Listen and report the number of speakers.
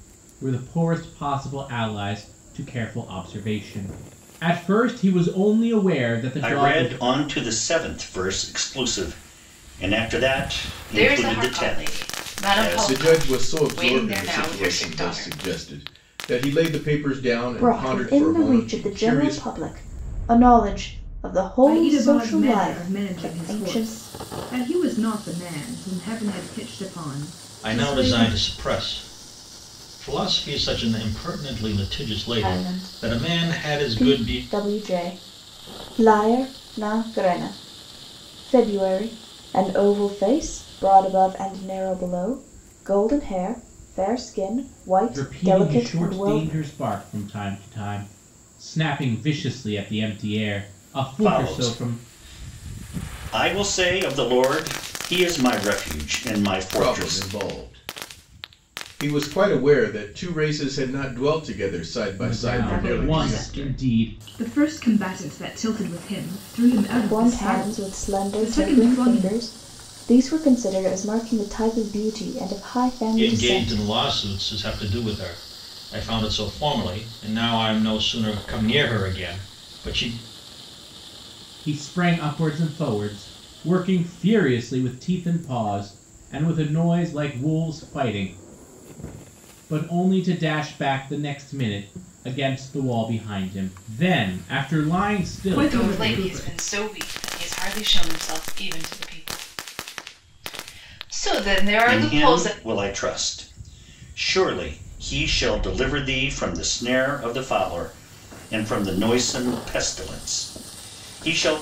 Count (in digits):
7